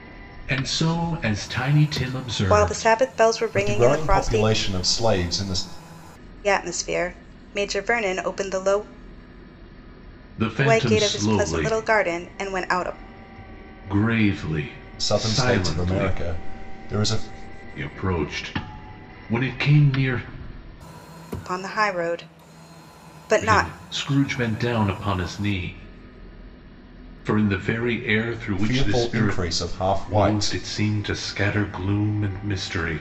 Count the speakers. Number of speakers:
three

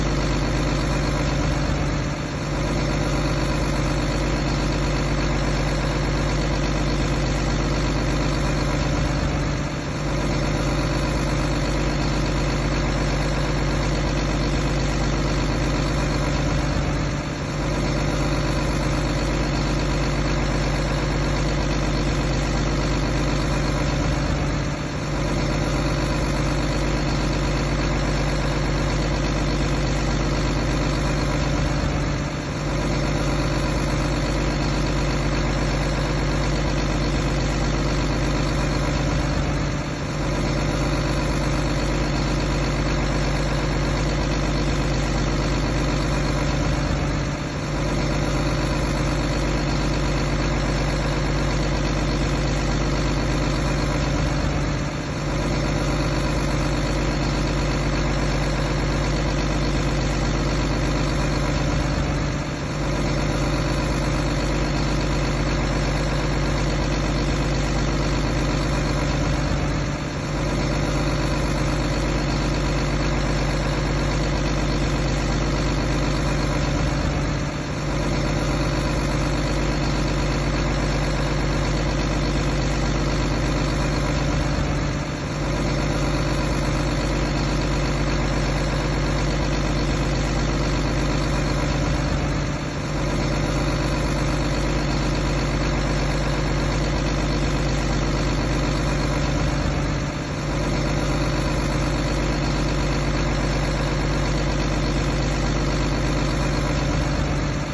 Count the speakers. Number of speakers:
zero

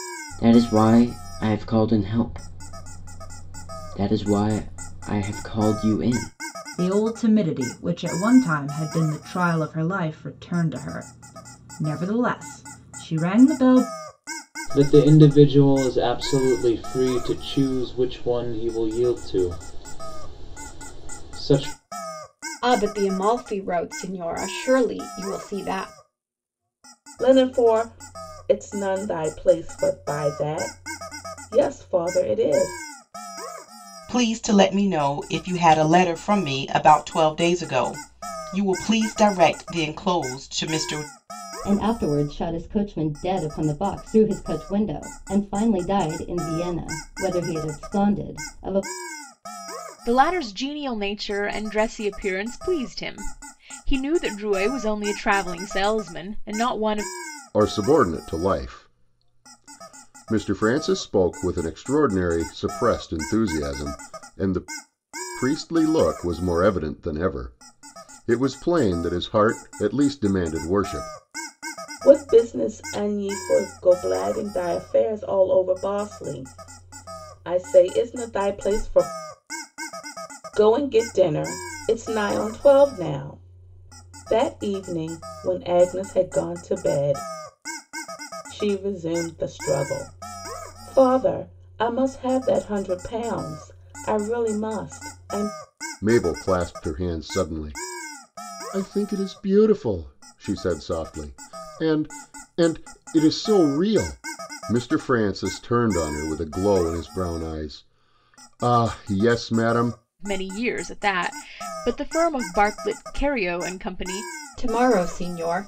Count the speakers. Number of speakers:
nine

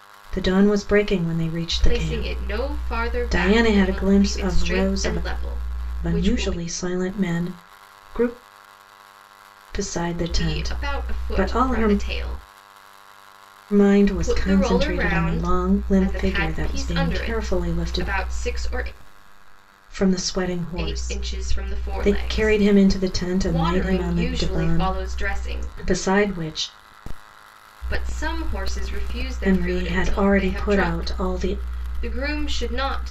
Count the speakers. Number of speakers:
two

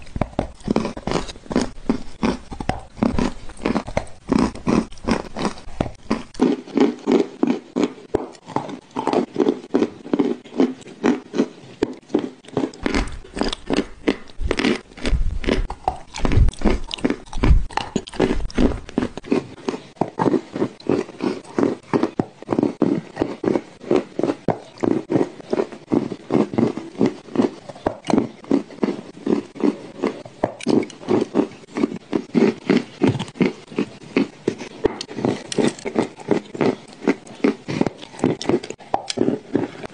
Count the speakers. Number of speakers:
zero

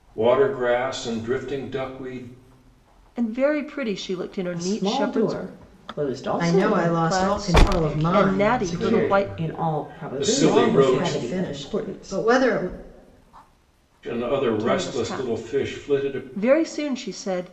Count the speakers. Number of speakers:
four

